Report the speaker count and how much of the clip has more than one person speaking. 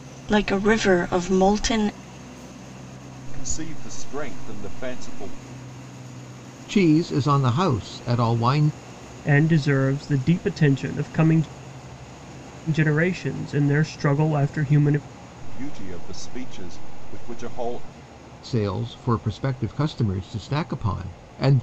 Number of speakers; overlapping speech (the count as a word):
four, no overlap